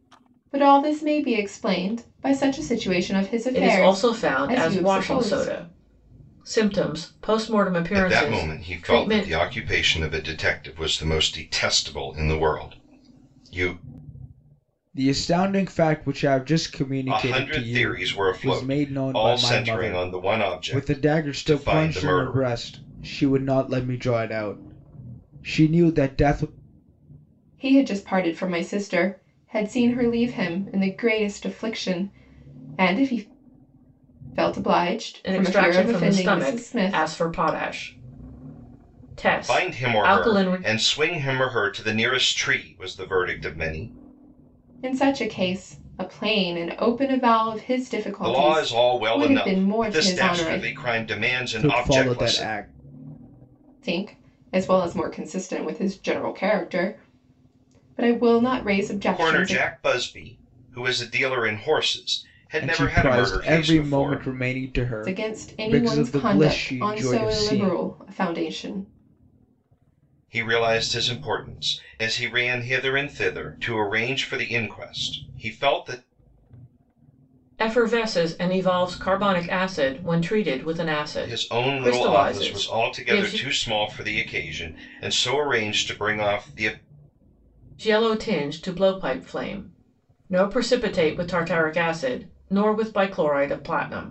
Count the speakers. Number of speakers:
four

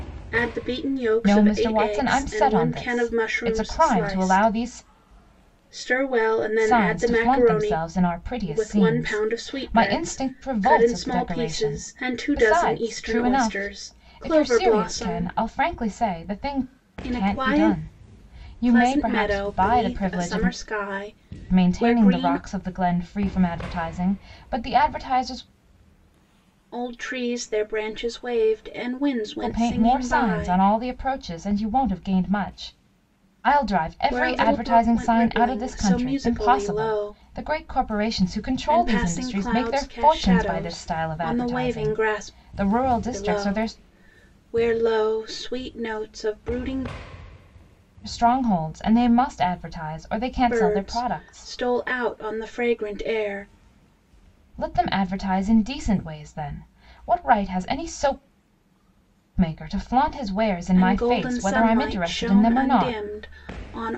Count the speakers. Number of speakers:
two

